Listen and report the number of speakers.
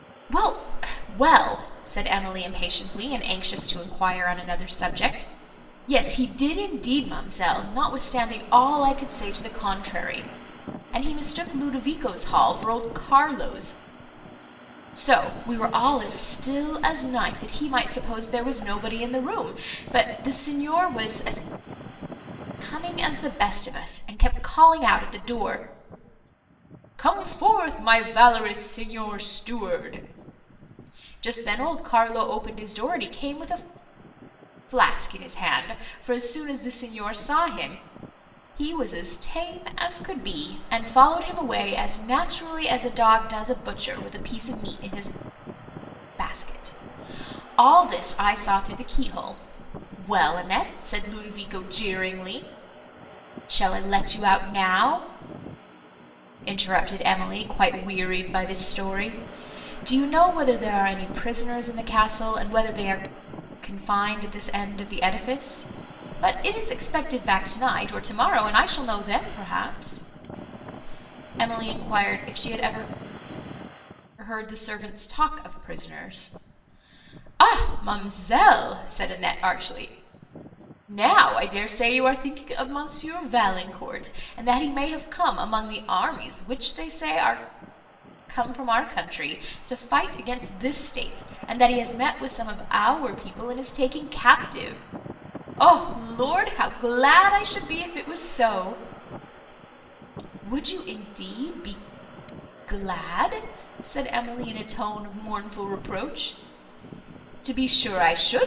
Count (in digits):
1